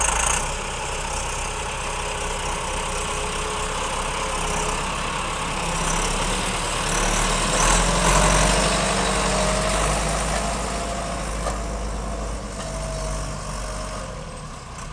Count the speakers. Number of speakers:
0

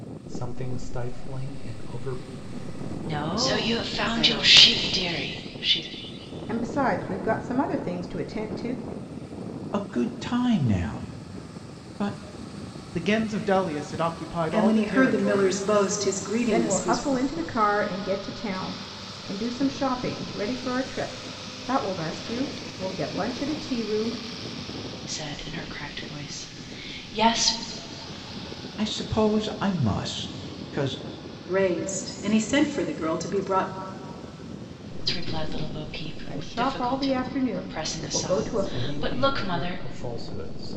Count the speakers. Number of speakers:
7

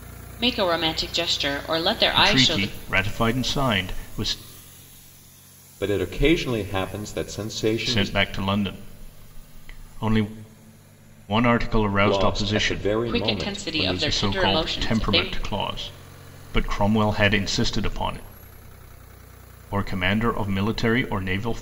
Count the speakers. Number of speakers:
3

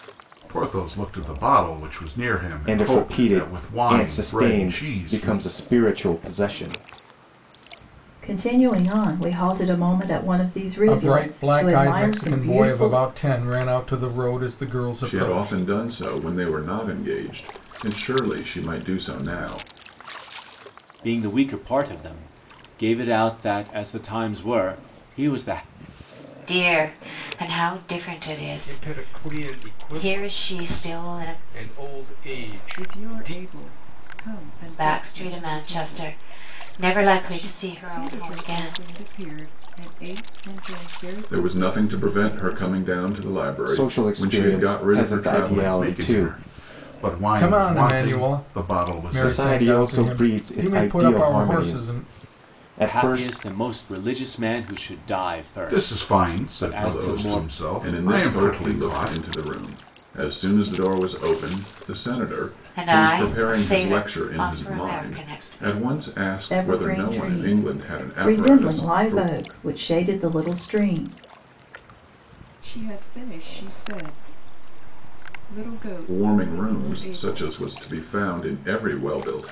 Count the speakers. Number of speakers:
9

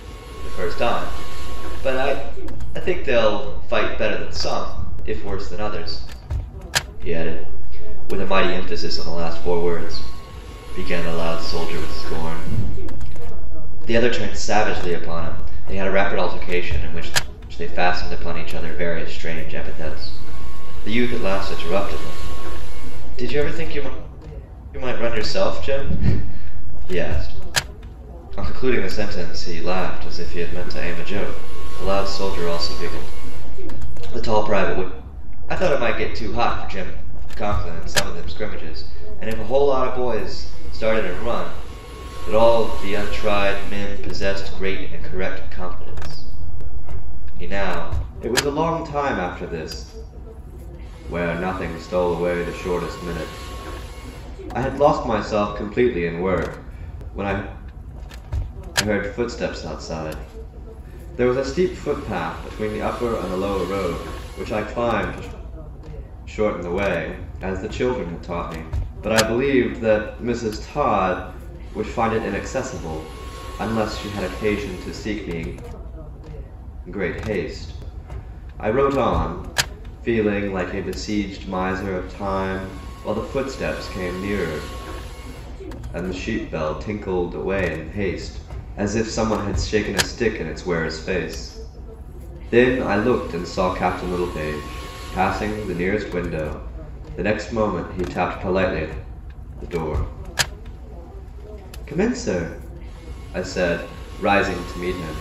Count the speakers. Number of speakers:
1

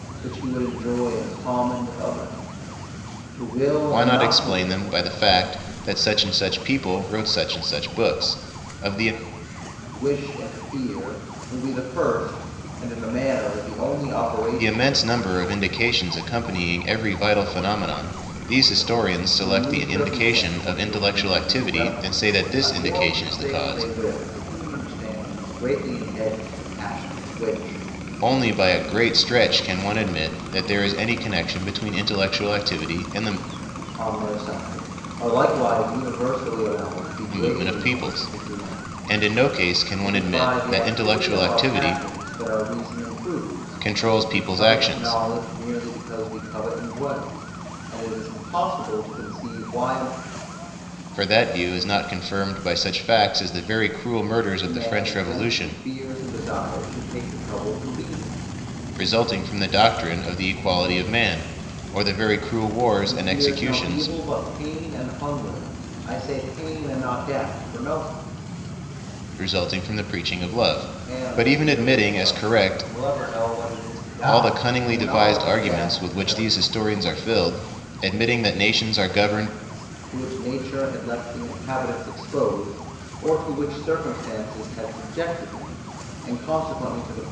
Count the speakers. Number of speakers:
2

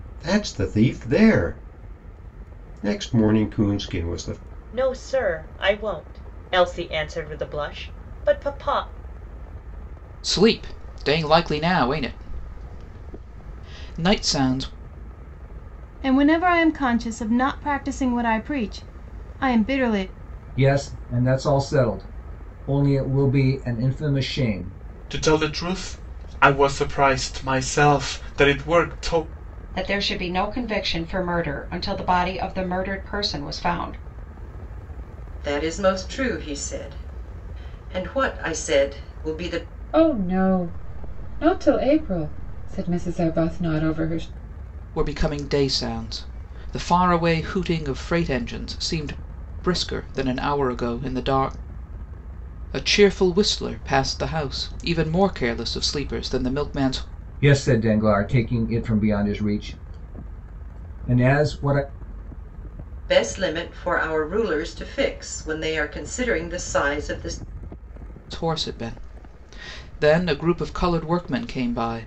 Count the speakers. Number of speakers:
9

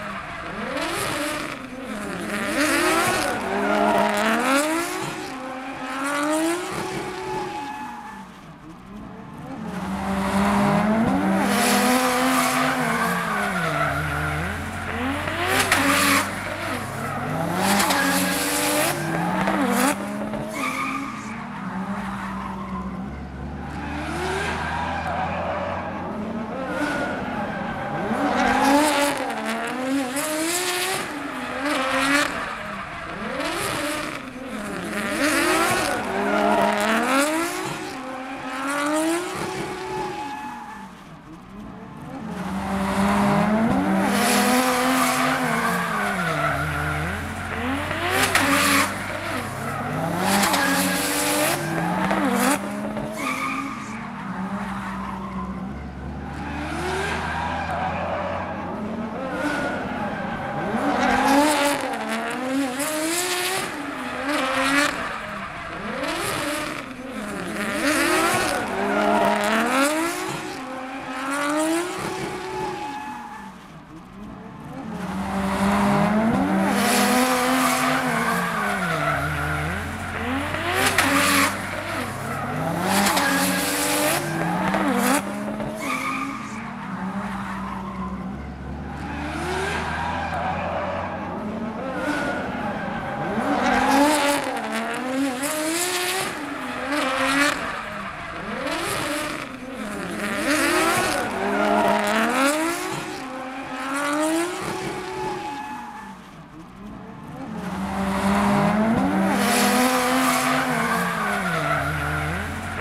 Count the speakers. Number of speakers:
0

